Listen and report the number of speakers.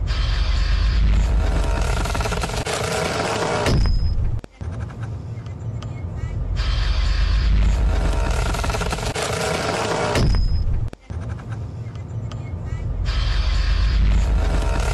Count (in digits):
0